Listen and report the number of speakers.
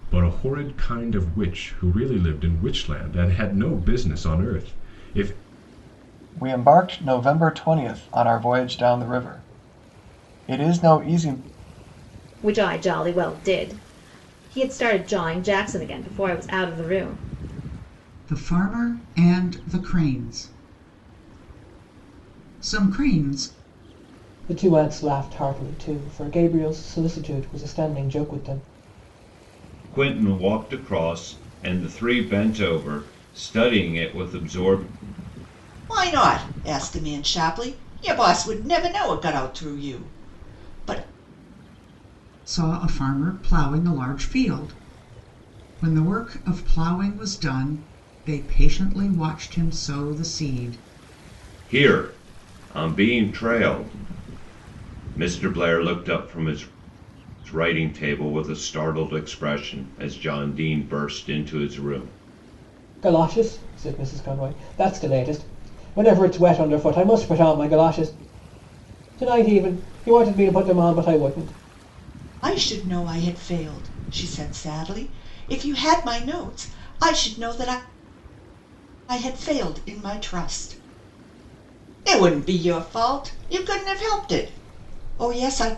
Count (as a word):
seven